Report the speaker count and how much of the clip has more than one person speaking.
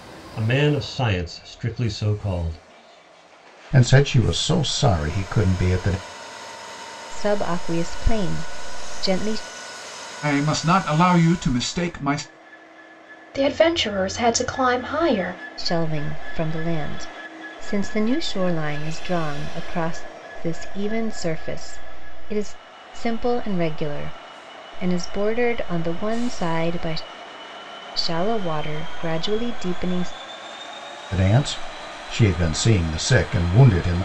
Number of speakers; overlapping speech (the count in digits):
5, no overlap